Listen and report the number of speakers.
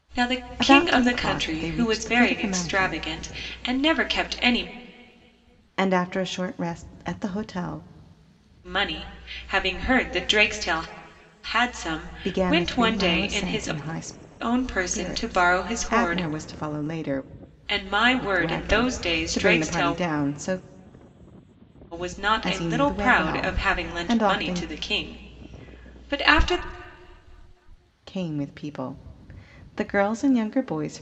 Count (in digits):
2